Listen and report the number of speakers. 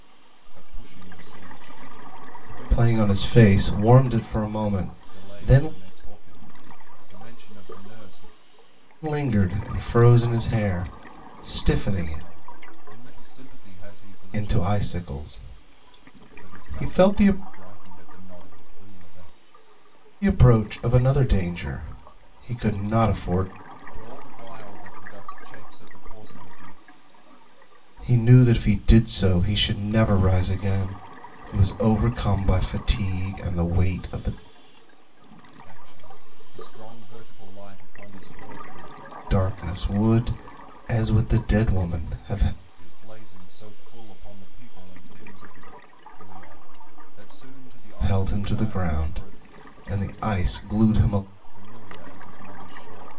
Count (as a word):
two